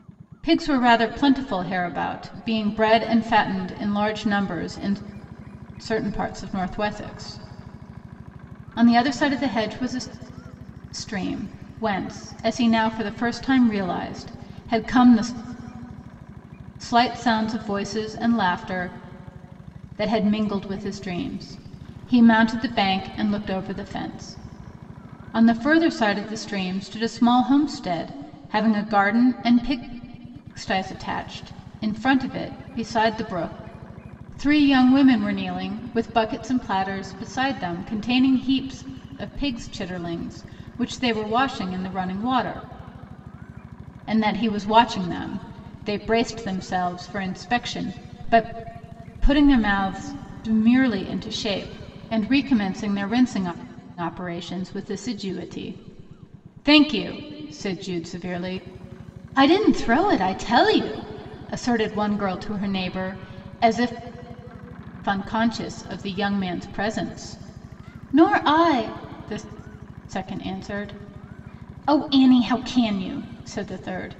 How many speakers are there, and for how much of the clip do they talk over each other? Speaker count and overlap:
1, no overlap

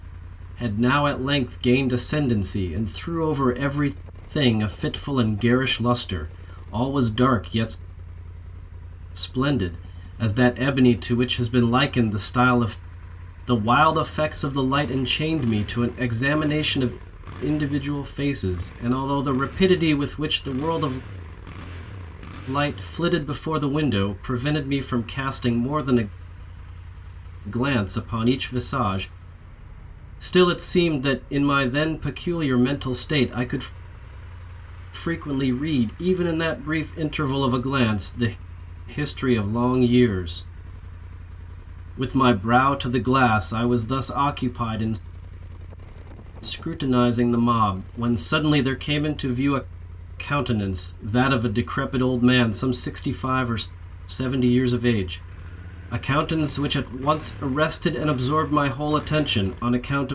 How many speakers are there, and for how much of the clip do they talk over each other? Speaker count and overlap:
1, no overlap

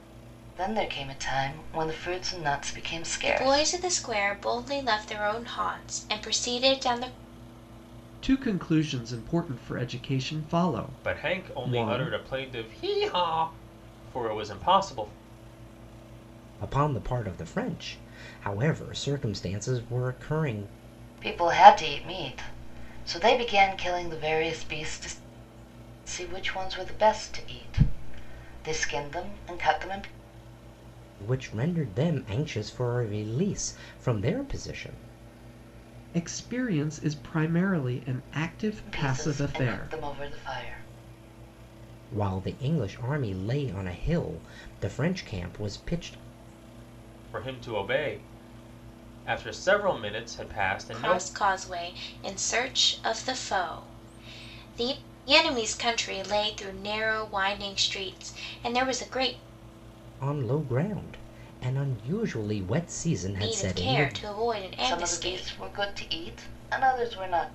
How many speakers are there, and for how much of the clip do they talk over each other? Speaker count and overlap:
5, about 7%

